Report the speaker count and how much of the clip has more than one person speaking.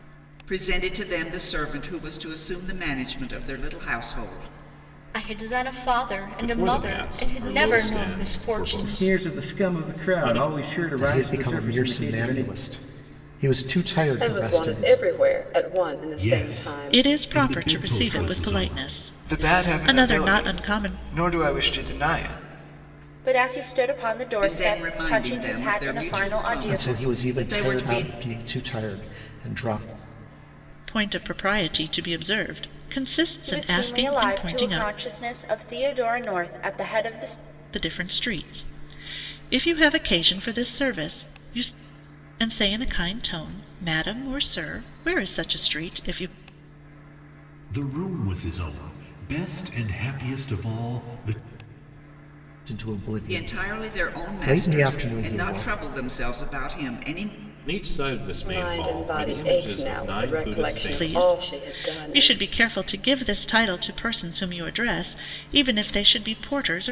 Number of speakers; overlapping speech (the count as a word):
ten, about 34%